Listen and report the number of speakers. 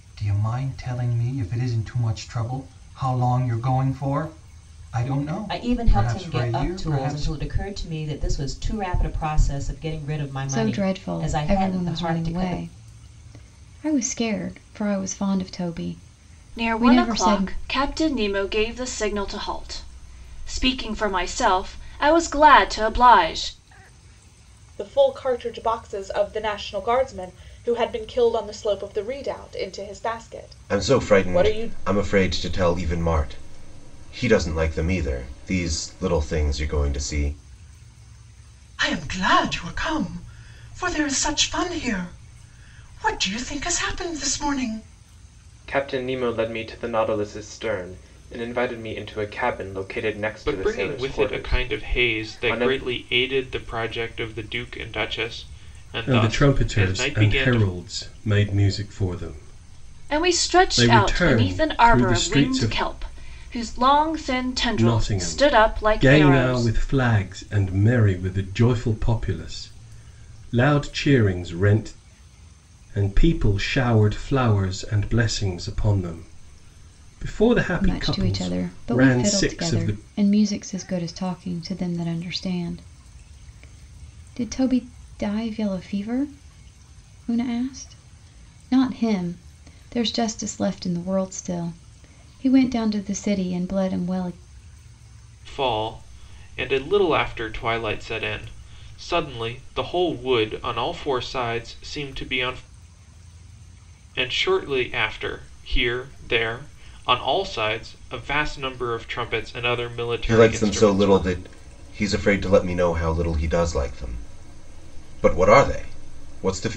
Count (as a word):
ten